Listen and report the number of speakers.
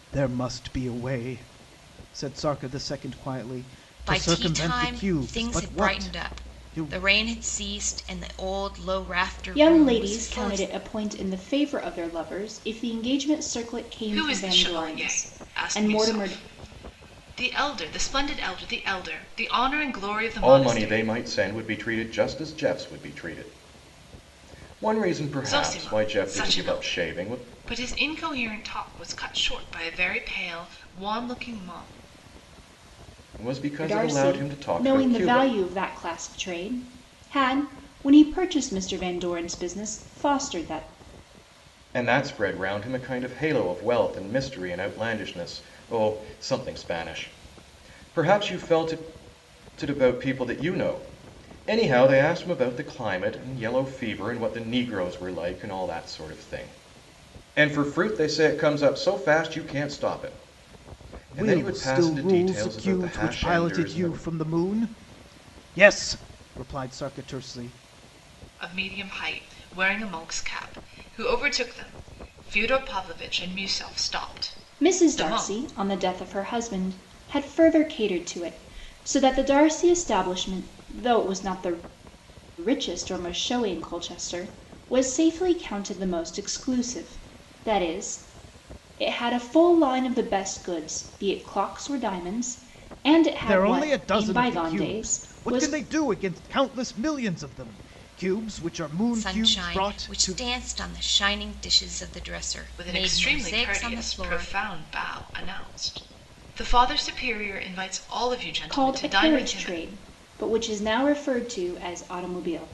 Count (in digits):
5